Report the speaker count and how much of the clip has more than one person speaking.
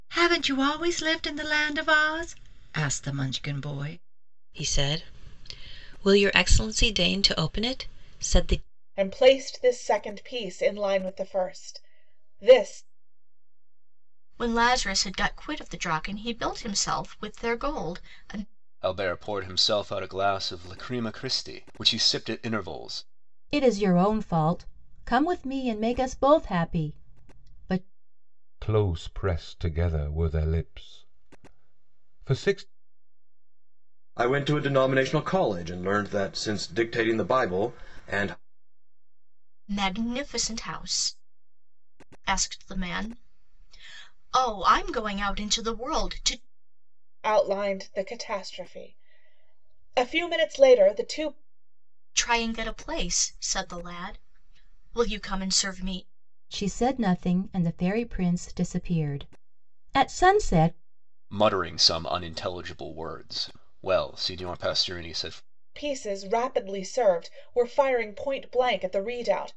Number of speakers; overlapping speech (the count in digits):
8, no overlap